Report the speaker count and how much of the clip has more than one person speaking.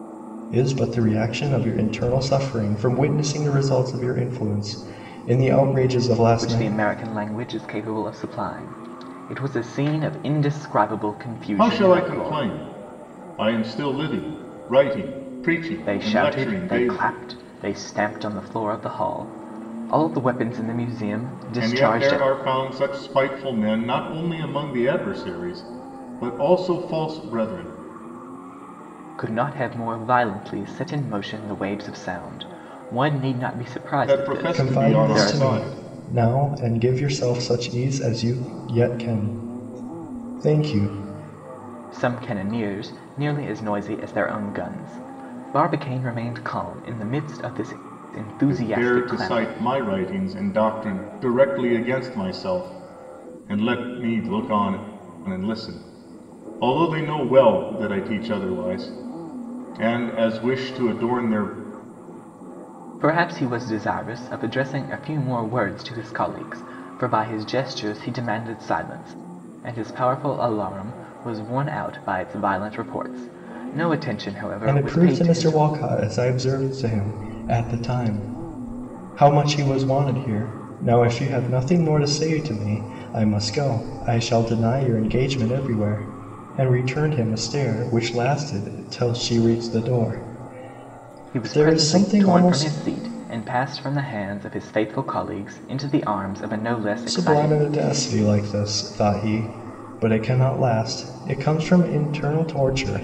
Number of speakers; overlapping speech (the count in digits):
3, about 9%